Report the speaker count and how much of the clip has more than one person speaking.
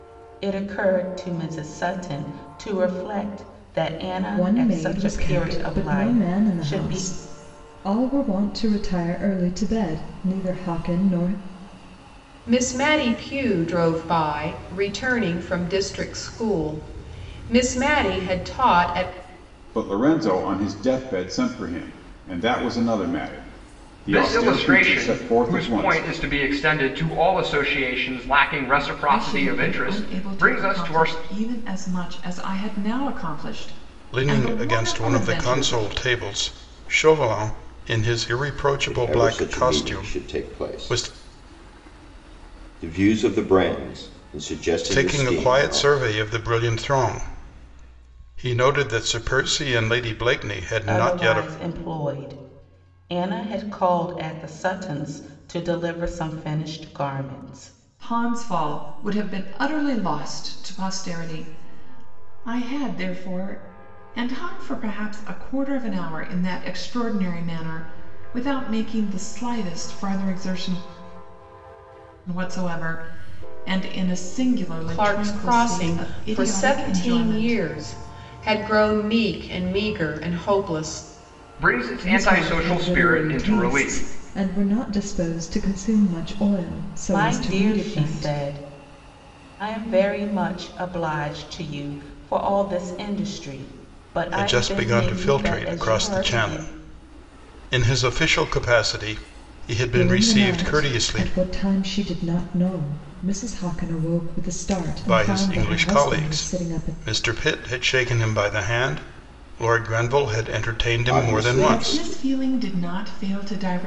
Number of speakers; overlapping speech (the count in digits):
8, about 22%